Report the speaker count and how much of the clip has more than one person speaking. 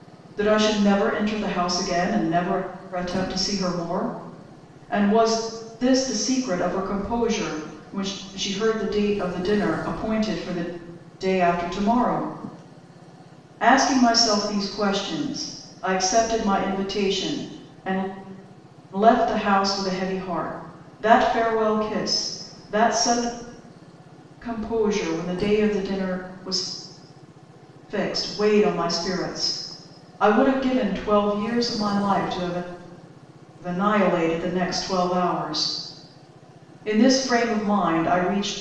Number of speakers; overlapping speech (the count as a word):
one, no overlap